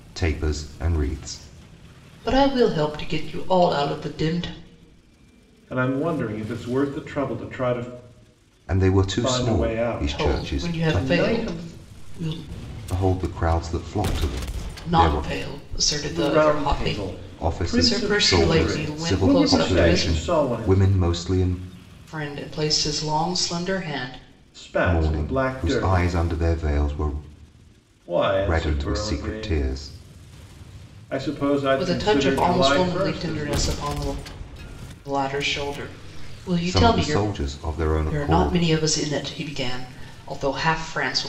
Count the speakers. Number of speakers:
3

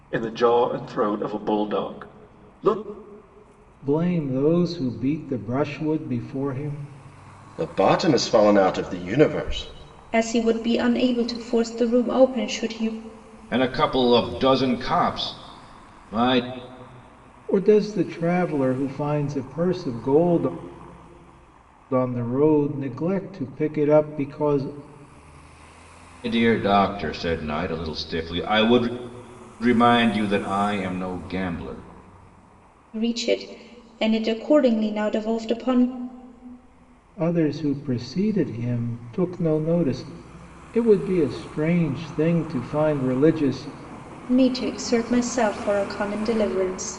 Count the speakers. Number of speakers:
5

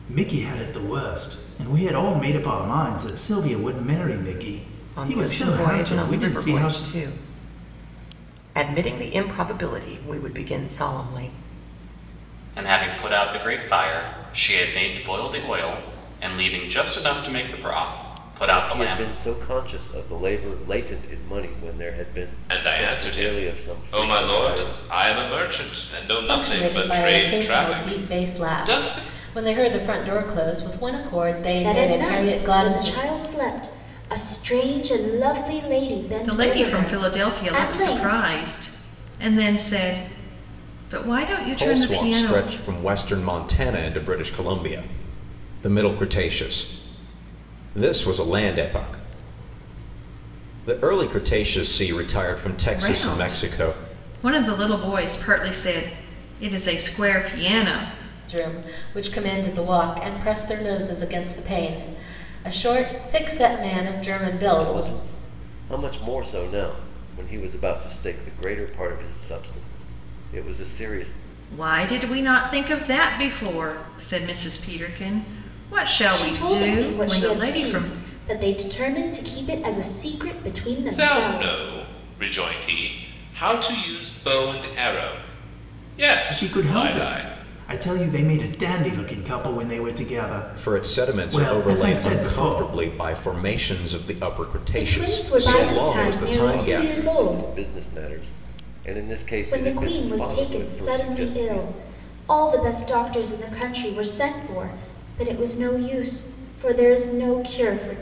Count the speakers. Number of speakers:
9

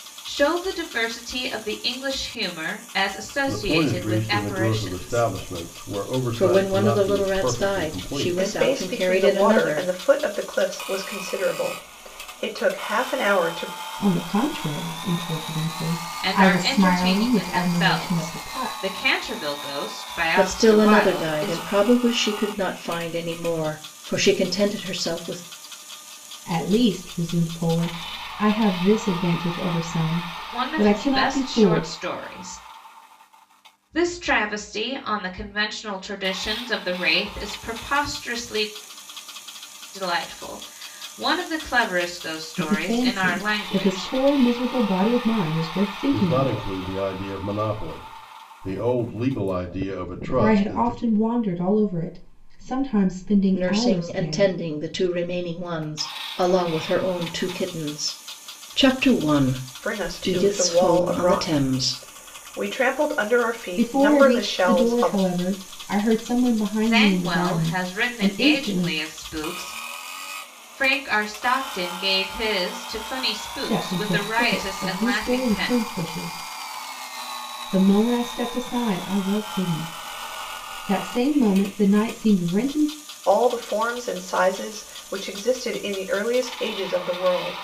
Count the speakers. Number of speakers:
5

